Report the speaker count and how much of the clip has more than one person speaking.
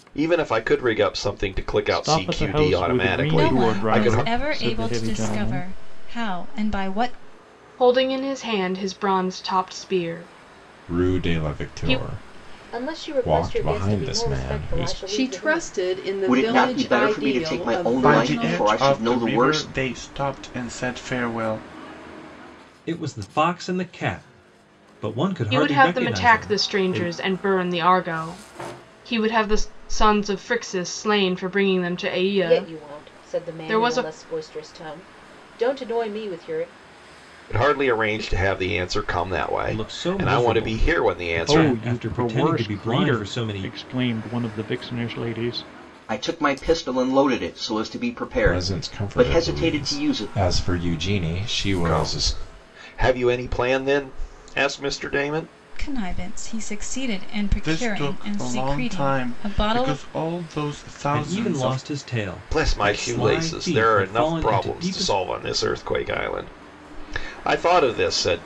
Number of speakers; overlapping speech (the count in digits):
10, about 41%